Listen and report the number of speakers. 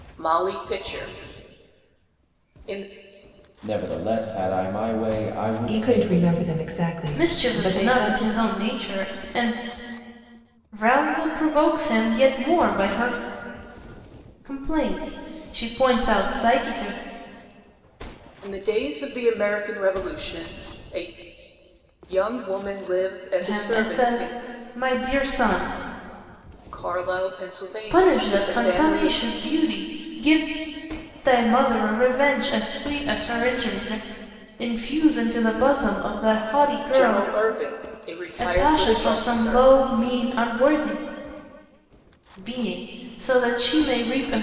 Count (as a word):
four